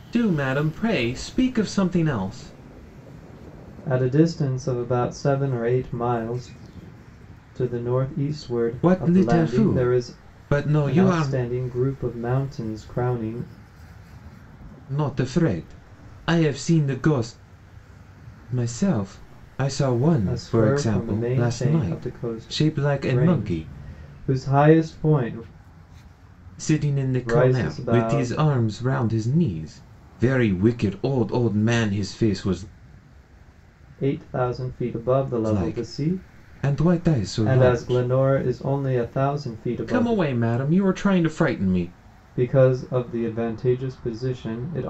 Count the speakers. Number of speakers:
2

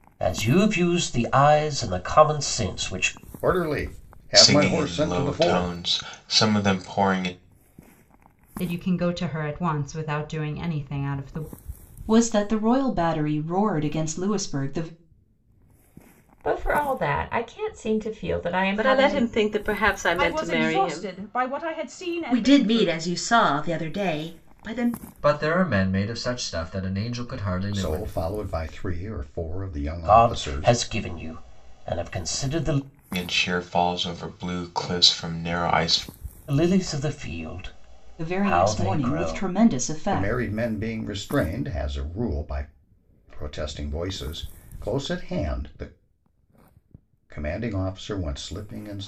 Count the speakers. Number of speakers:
10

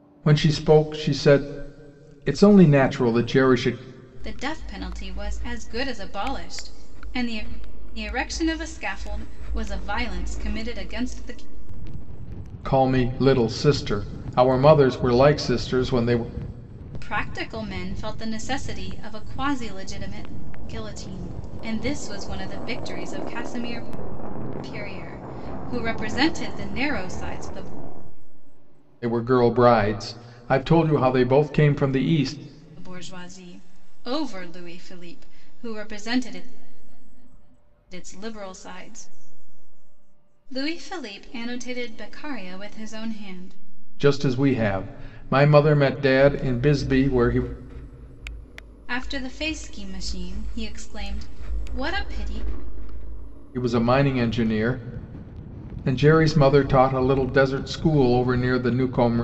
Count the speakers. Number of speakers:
2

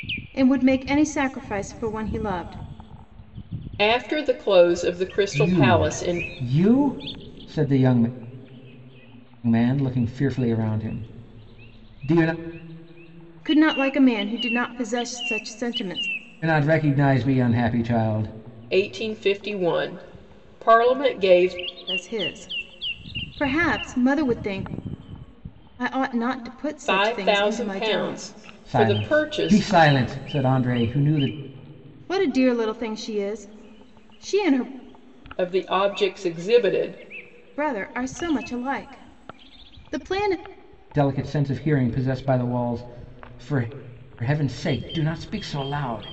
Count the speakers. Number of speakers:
3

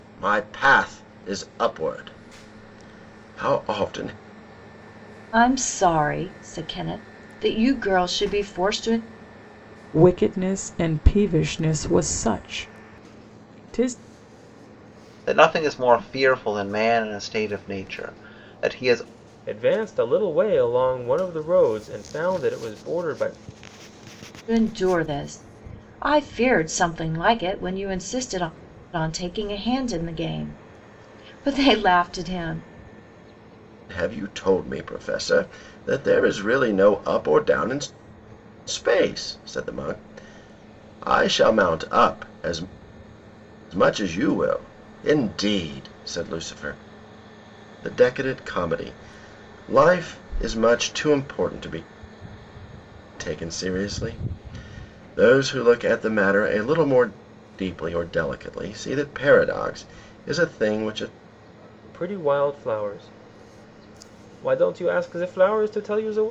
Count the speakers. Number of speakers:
5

